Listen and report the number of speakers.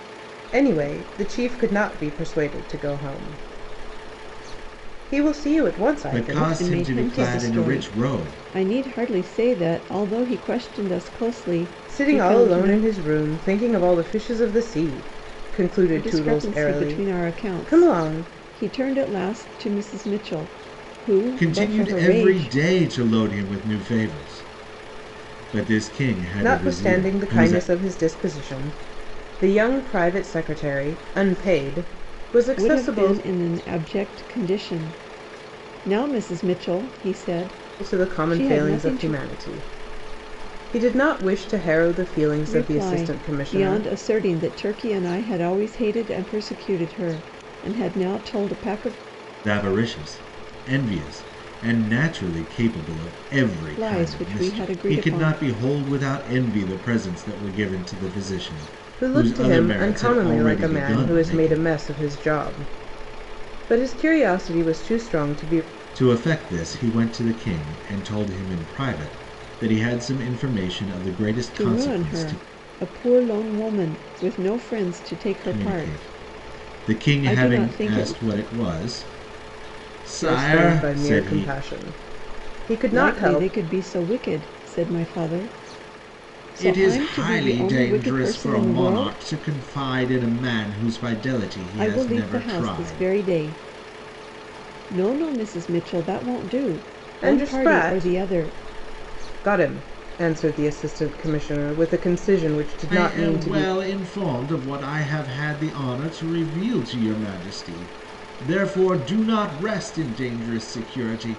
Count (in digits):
3